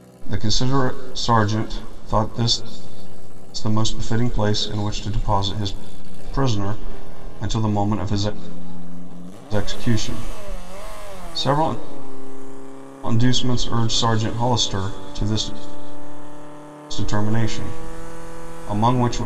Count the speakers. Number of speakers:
one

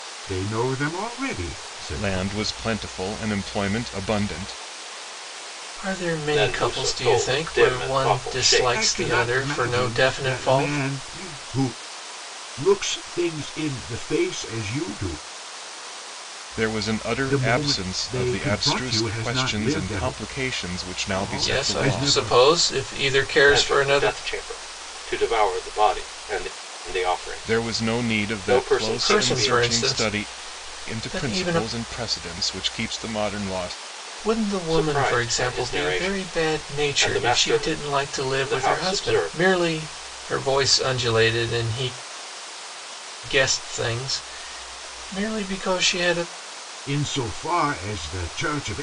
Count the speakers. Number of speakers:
four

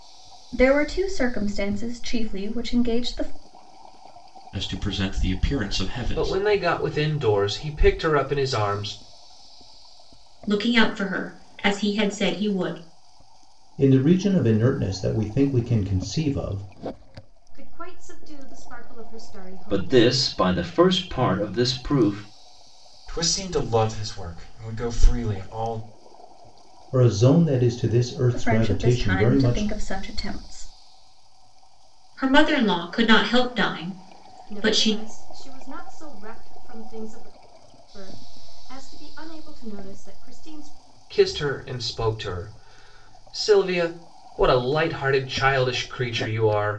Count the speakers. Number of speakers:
eight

